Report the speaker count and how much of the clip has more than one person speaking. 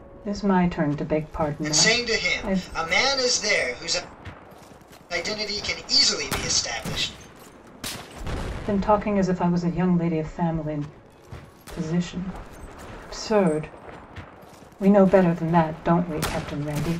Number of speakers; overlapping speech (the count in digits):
2, about 7%